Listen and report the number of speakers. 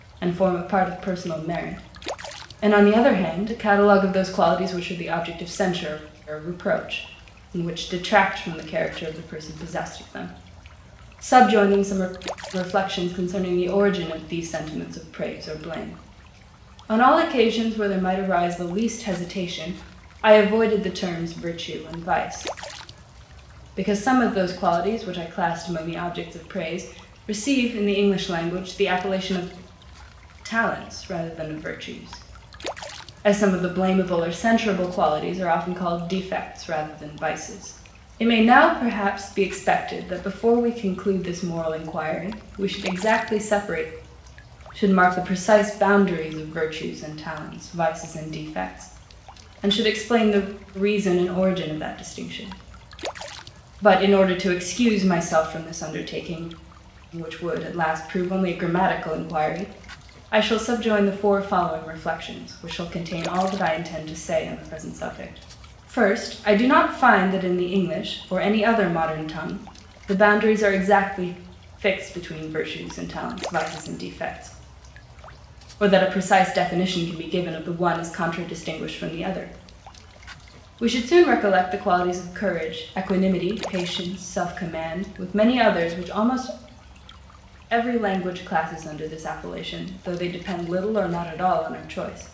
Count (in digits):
1